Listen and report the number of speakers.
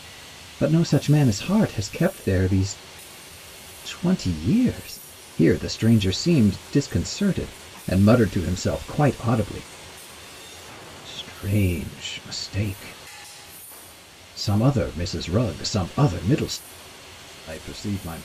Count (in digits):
1